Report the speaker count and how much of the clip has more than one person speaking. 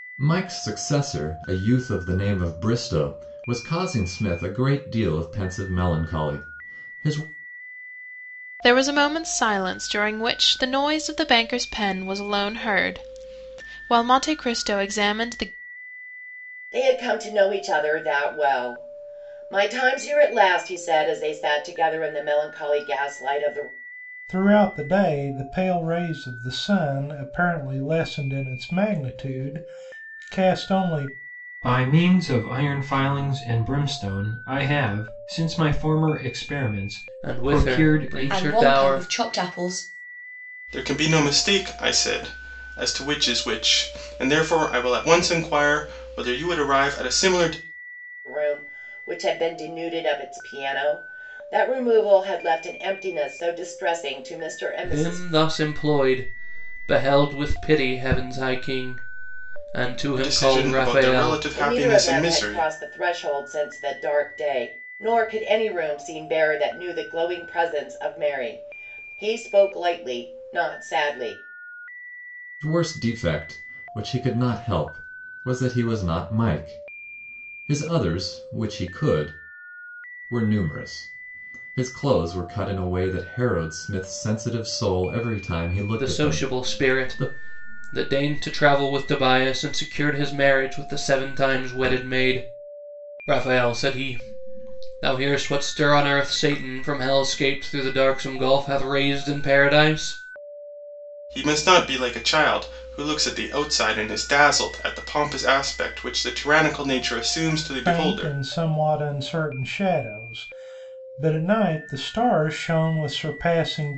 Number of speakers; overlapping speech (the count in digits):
8, about 6%